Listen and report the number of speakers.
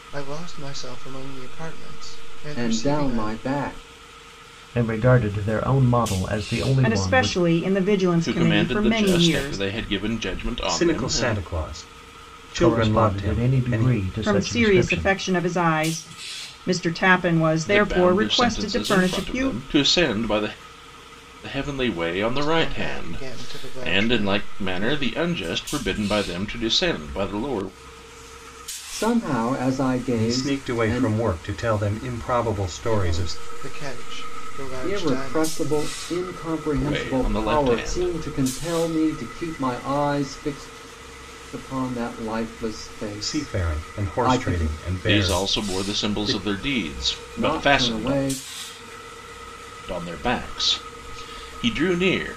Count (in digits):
6